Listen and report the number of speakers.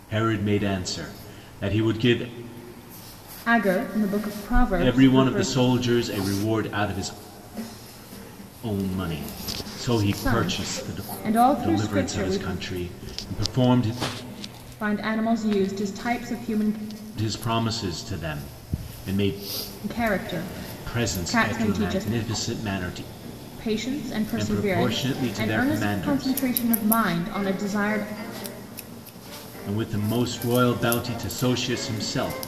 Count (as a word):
two